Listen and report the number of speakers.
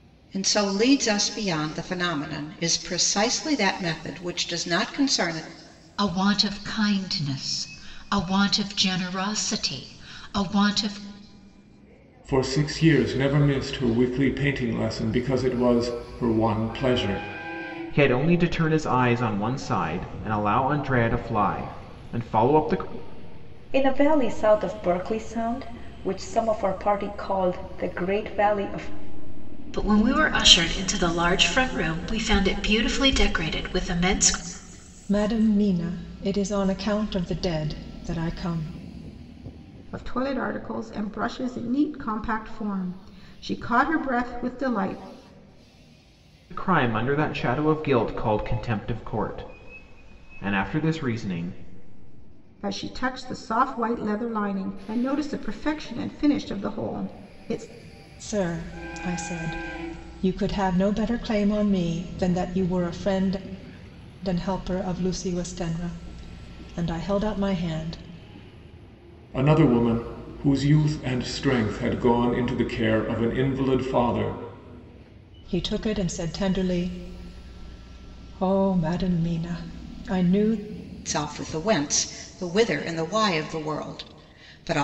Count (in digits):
8